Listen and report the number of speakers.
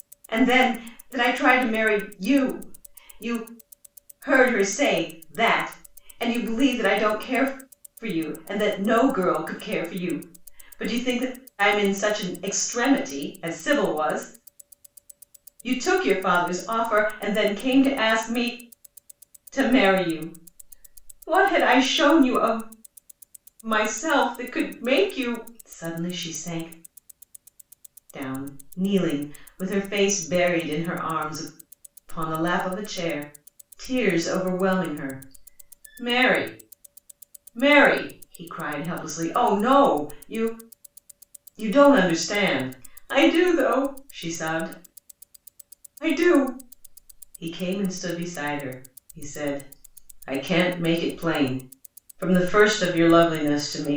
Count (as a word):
one